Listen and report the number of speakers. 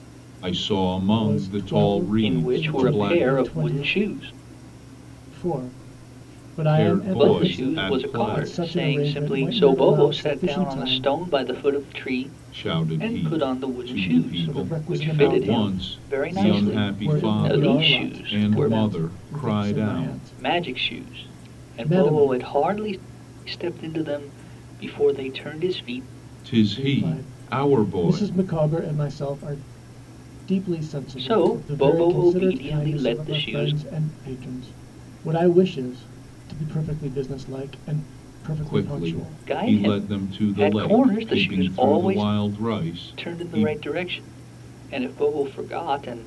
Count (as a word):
three